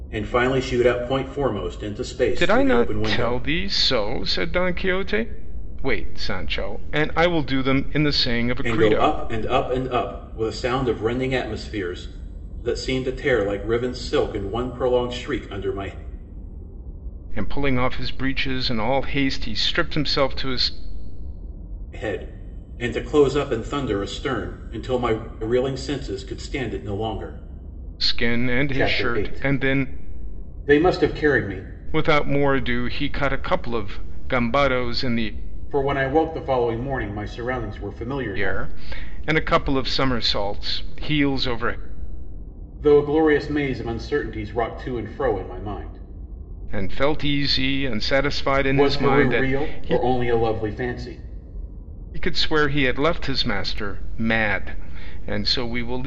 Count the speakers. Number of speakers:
two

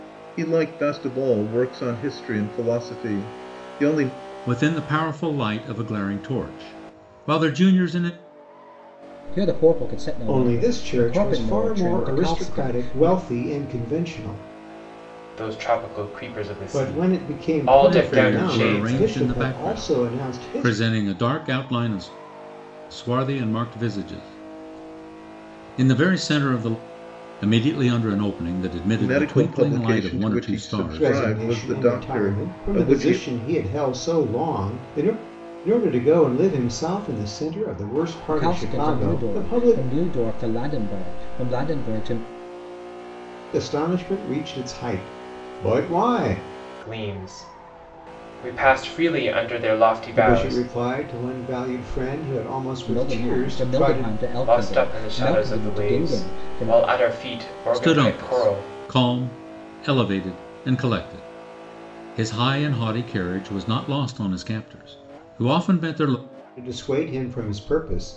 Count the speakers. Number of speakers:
five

